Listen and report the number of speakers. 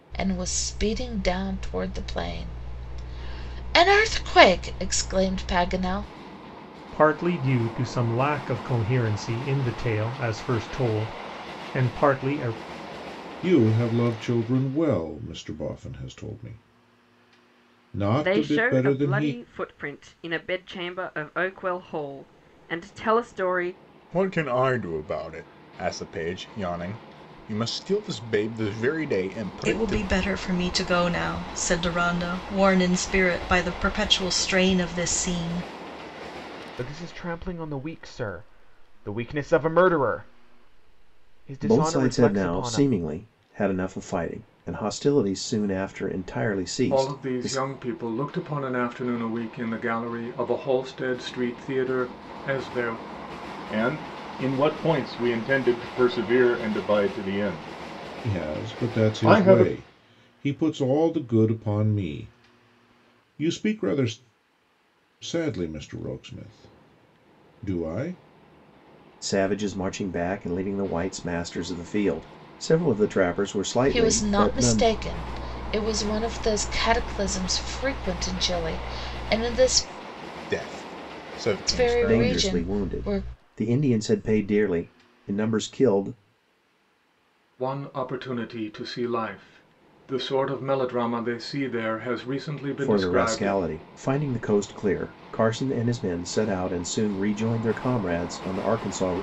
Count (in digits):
10